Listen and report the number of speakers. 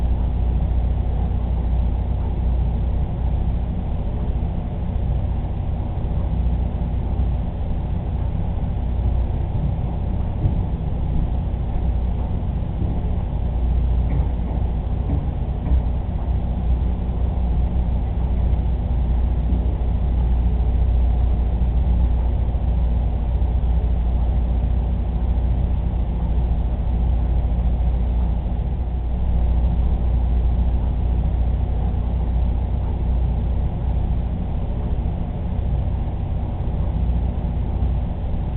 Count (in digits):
0